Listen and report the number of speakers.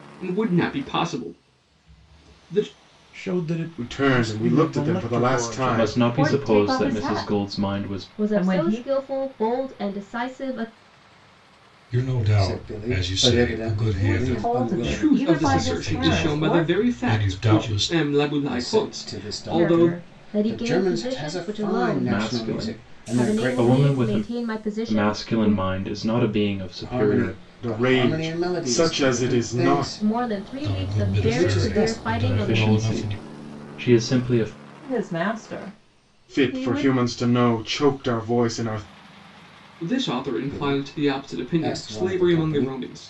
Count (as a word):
eight